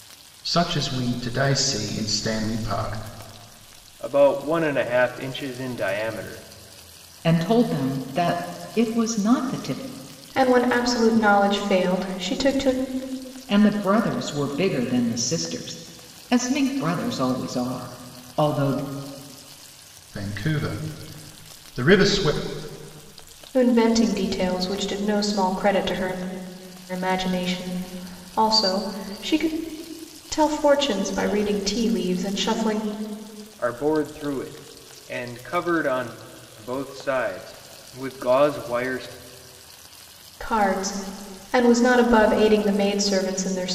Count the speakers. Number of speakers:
4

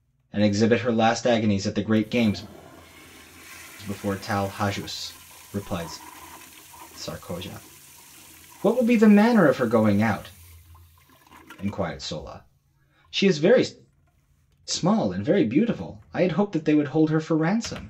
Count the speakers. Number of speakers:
1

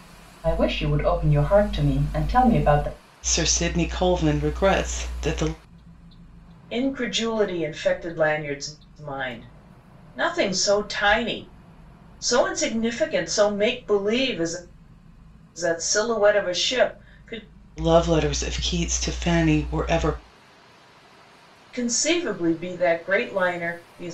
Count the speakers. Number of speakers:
3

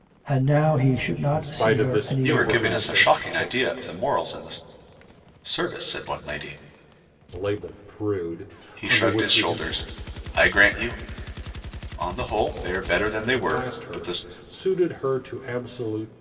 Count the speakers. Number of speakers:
3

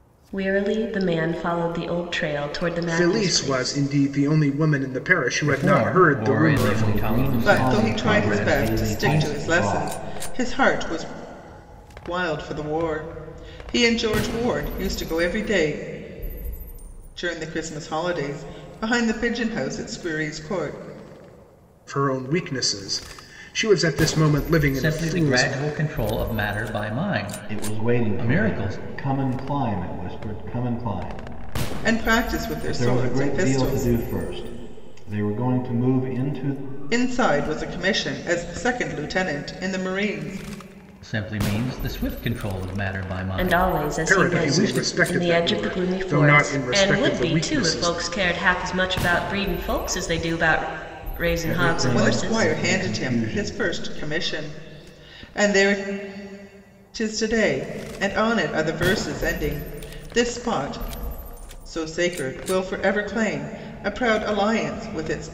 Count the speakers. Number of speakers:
5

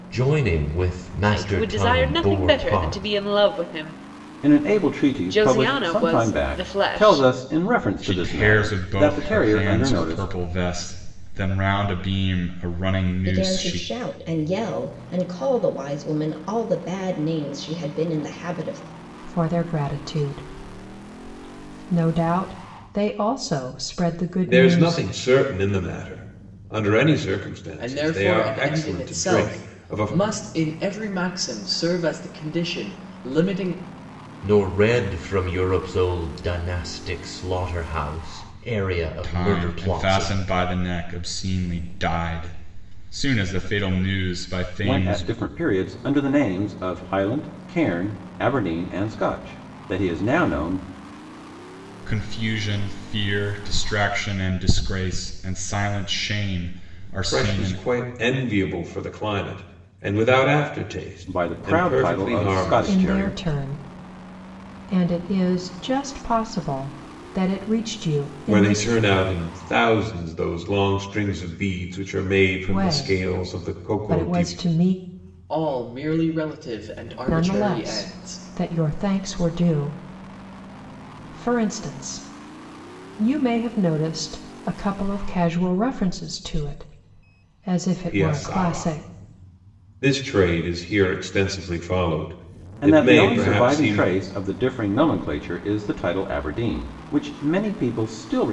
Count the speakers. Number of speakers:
8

